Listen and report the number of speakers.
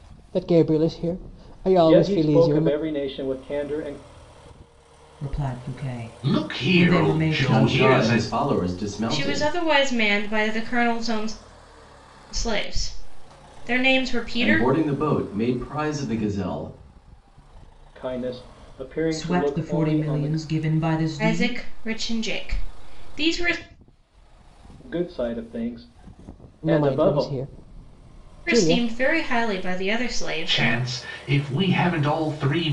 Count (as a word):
six